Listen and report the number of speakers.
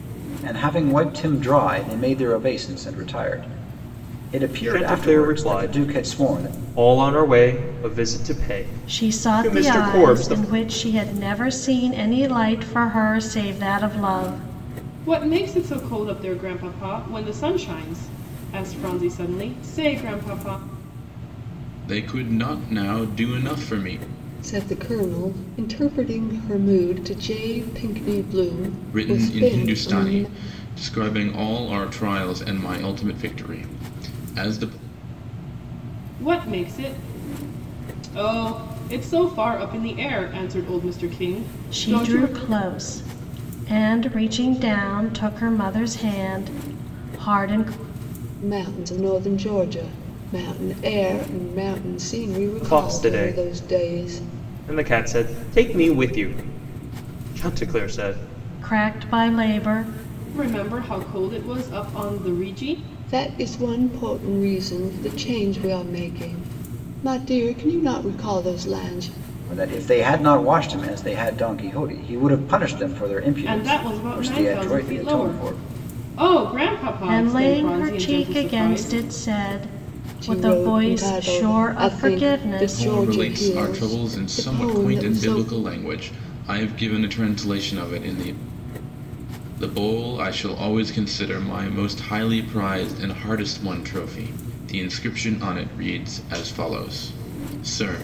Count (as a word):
six